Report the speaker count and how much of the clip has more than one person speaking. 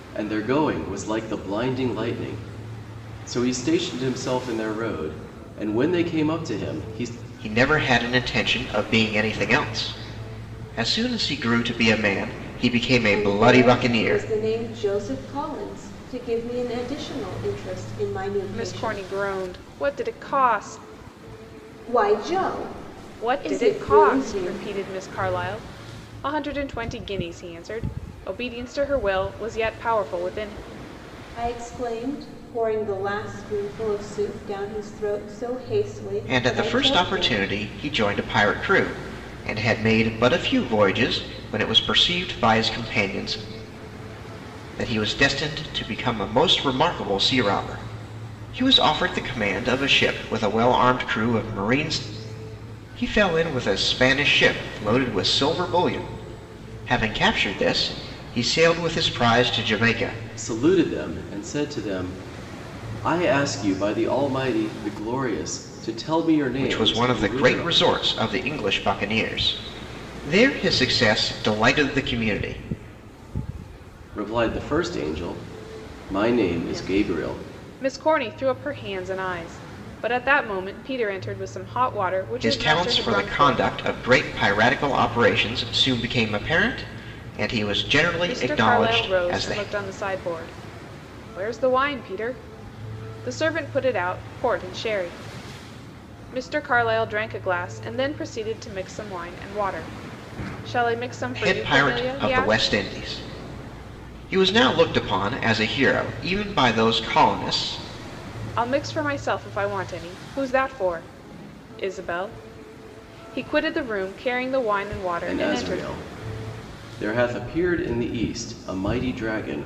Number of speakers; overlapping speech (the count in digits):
4, about 9%